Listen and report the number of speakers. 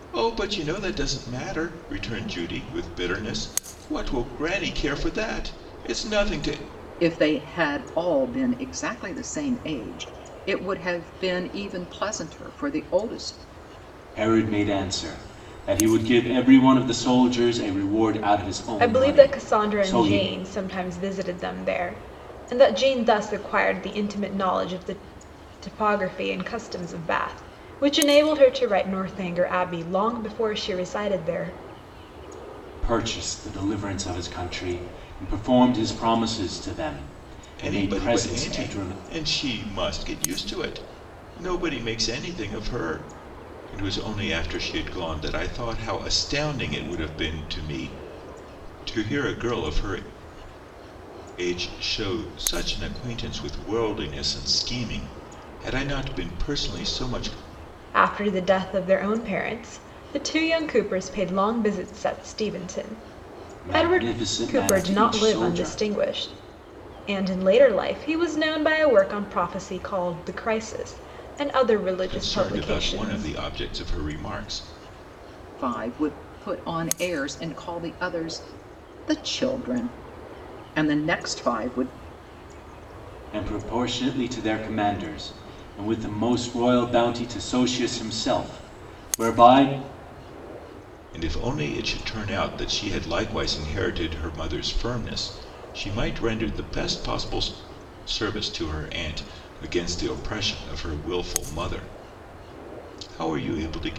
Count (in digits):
4